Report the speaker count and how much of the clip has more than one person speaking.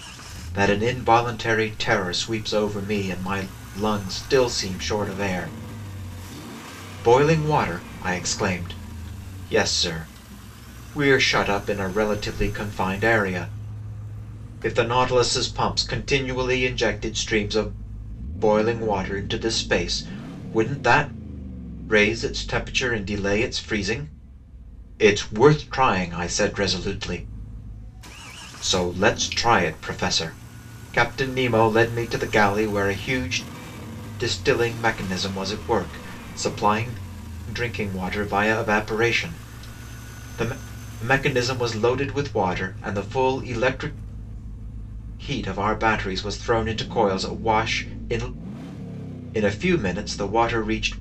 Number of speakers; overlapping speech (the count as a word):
one, no overlap